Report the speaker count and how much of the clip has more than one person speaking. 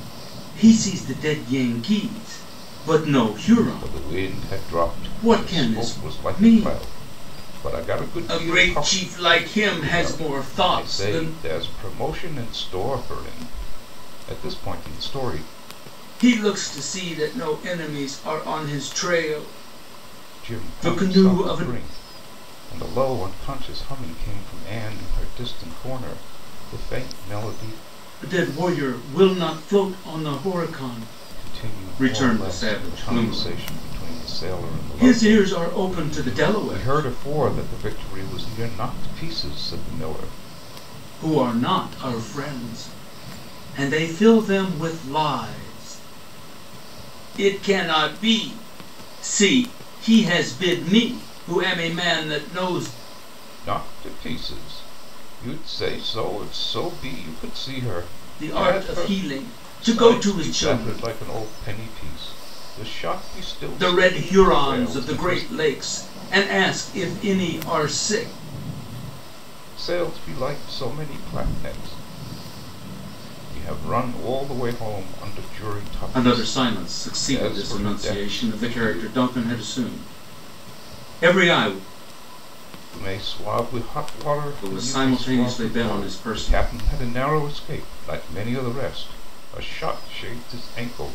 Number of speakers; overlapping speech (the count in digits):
2, about 23%